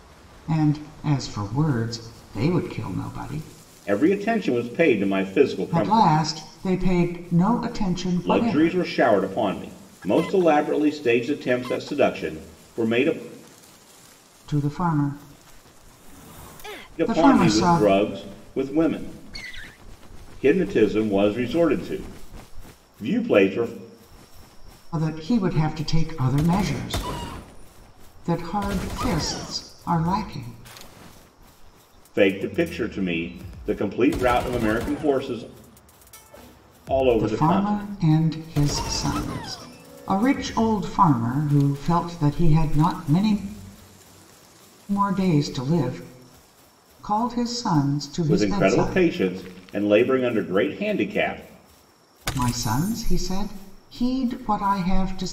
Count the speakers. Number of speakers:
2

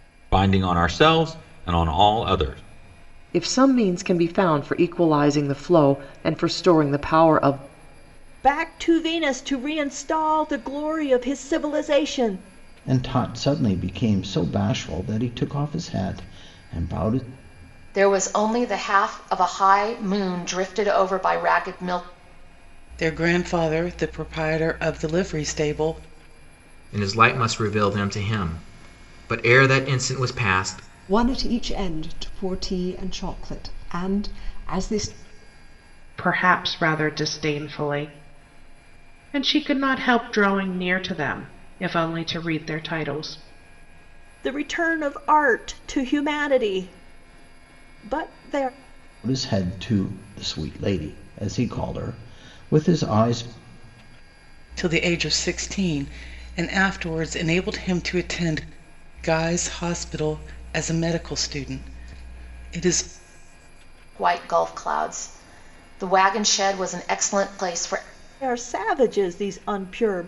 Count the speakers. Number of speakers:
9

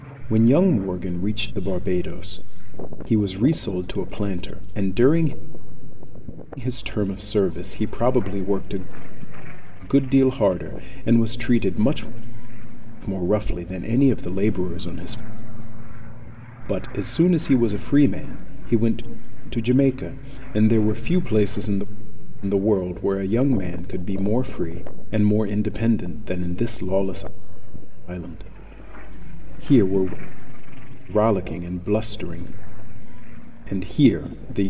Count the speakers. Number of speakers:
1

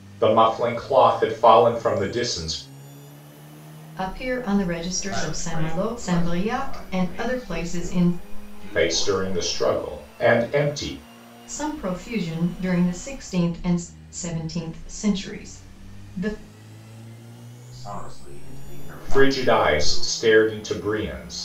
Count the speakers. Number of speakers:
3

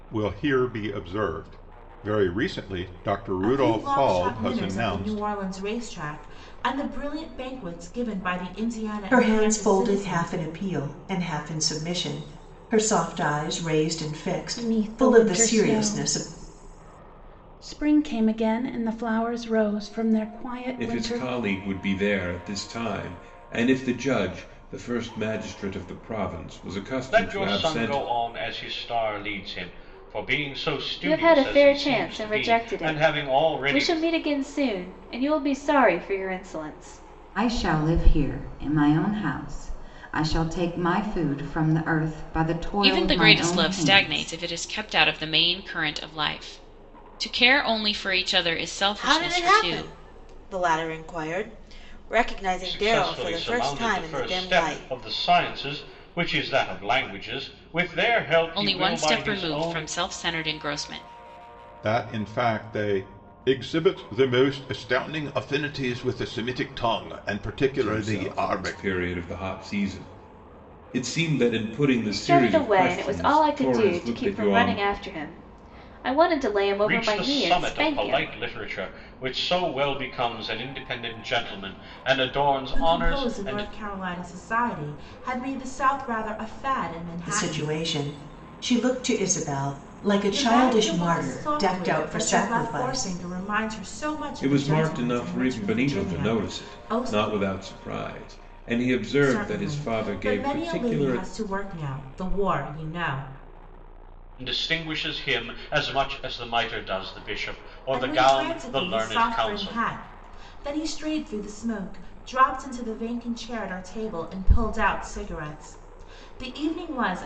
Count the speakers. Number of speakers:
10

